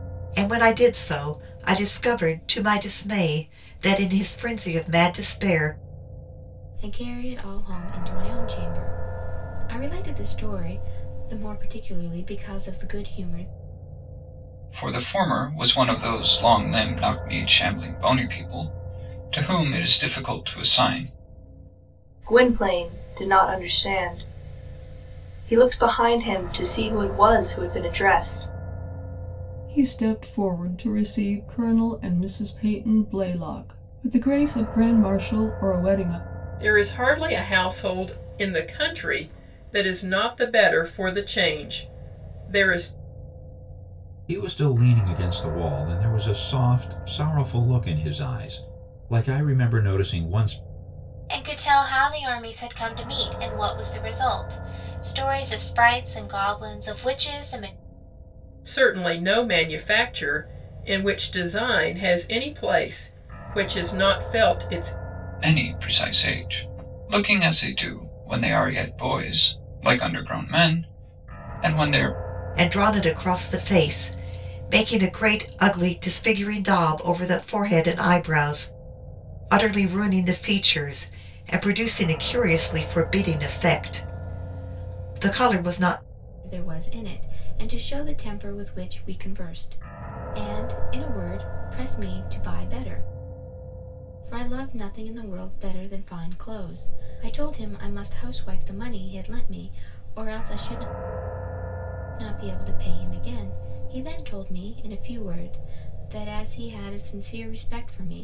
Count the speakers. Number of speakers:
8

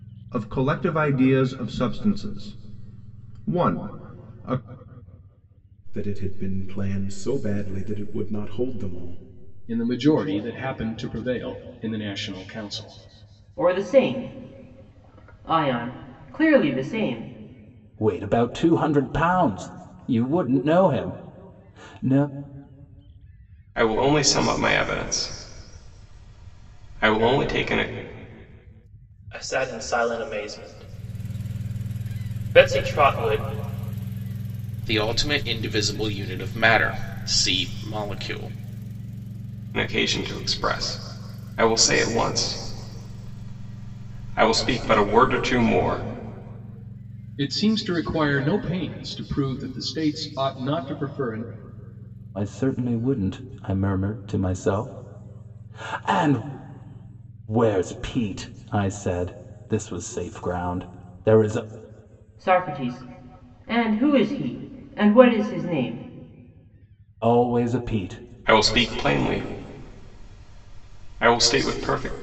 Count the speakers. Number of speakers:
8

